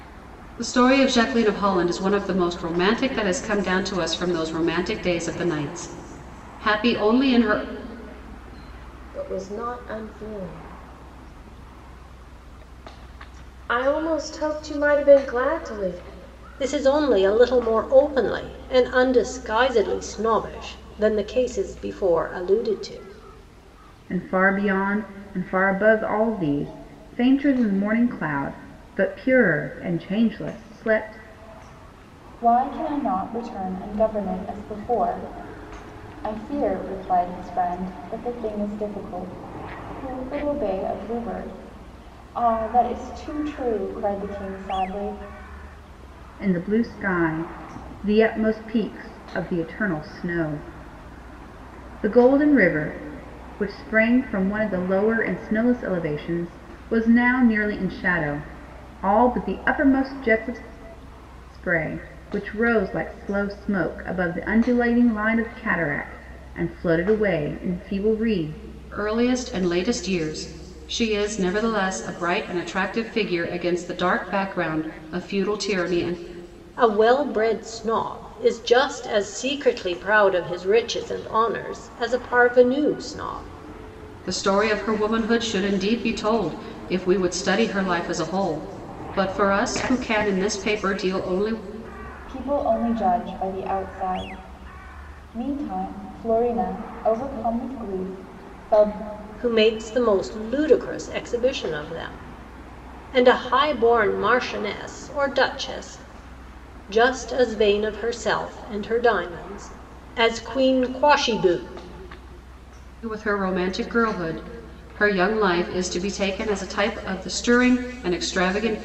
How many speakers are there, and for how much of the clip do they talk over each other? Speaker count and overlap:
five, no overlap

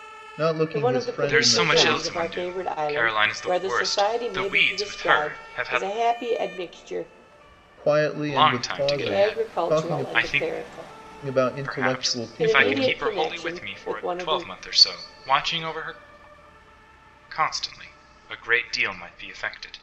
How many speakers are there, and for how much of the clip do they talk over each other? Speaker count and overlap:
three, about 52%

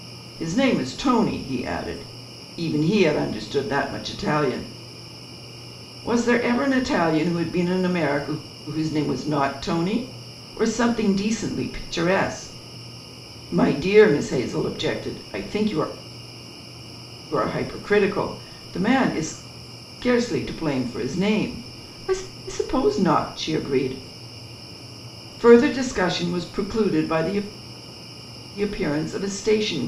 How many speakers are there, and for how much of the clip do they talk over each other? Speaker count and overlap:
one, no overlap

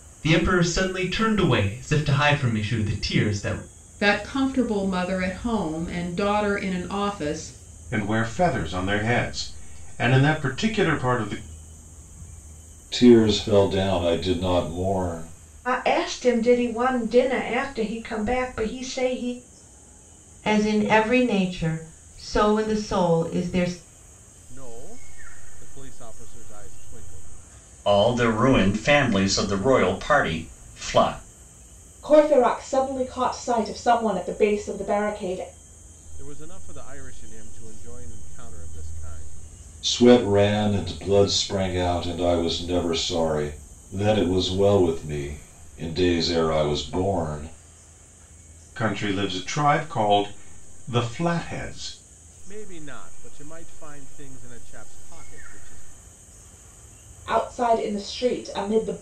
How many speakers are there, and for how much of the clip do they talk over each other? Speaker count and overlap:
nine, no overlap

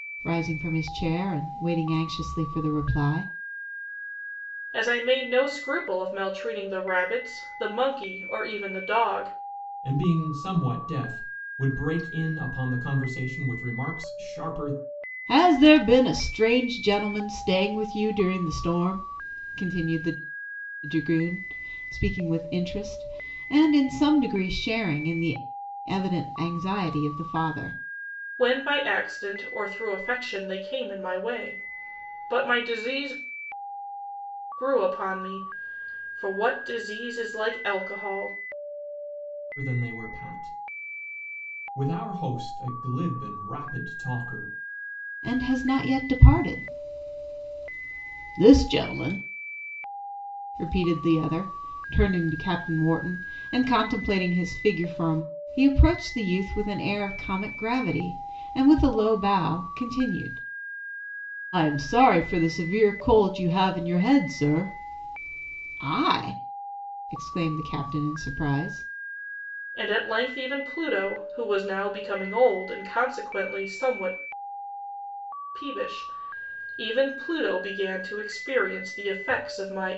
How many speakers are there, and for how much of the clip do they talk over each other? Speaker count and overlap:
three, no overlap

